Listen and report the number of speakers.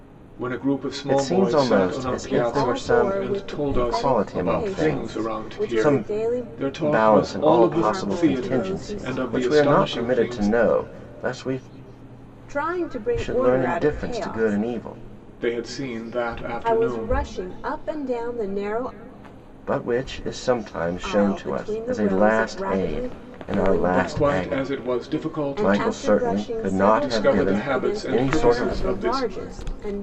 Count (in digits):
3